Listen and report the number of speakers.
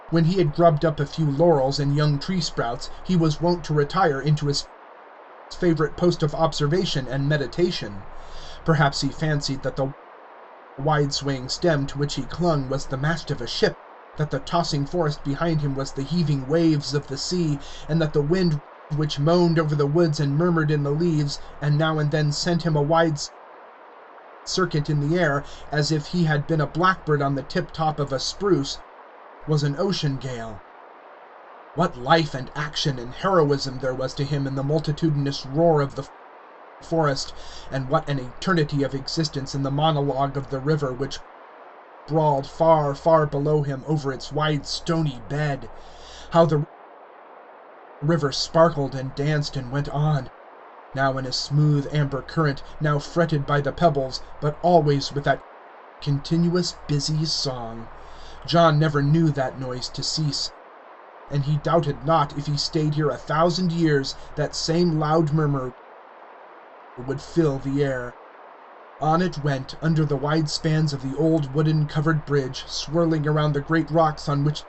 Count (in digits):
1